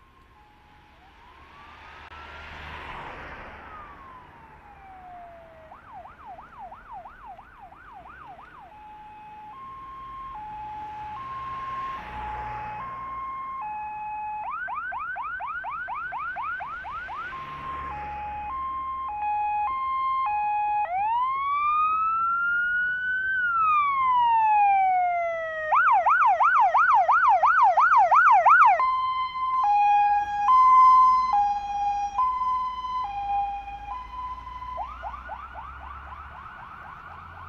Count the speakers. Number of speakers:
zero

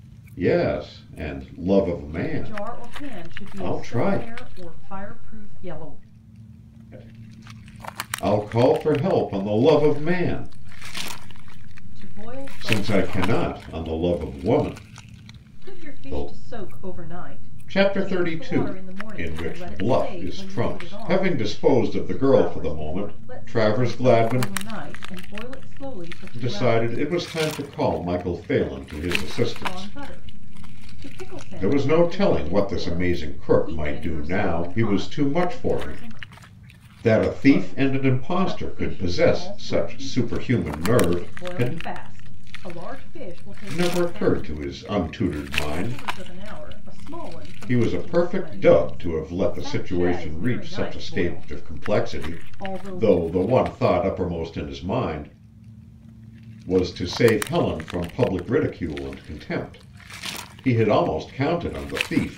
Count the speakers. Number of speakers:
two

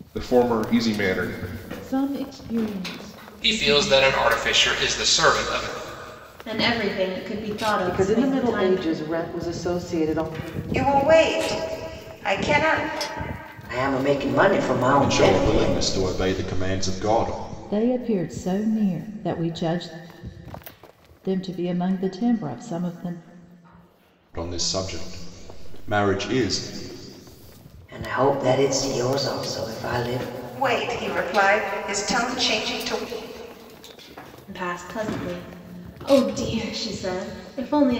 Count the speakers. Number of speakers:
nine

